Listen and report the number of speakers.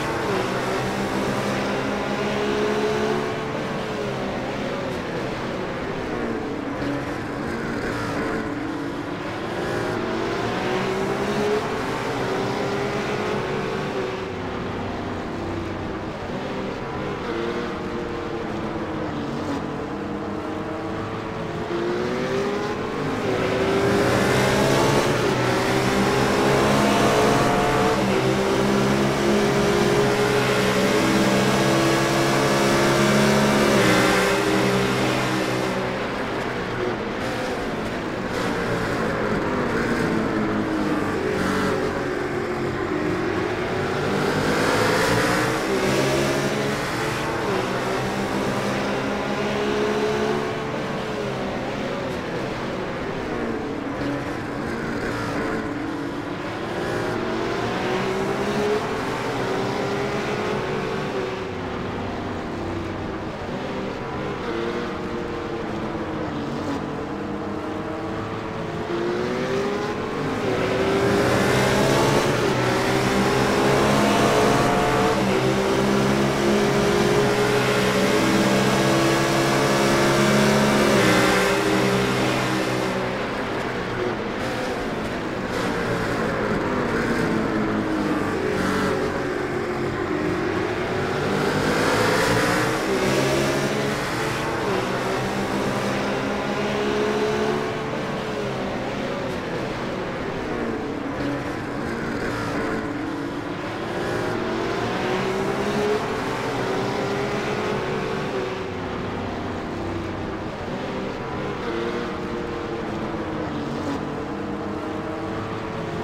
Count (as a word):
zero